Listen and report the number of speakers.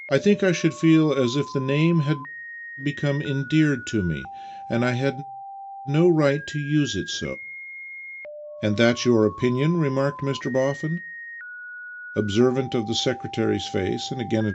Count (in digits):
1